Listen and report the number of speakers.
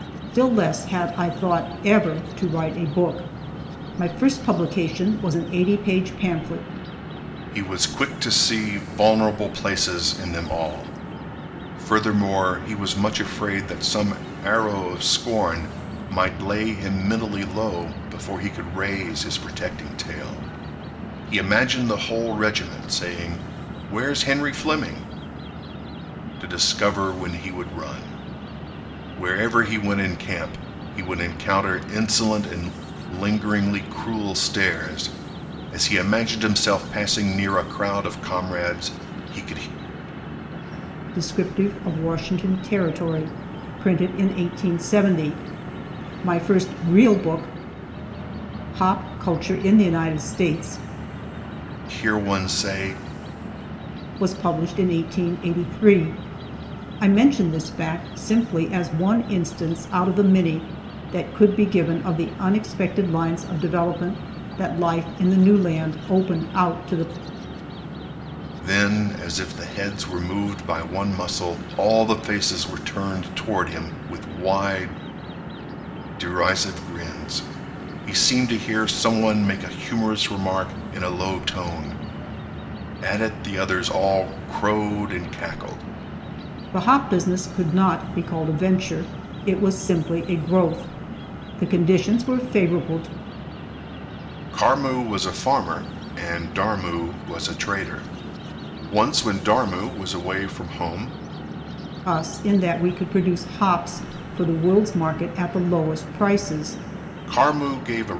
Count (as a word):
two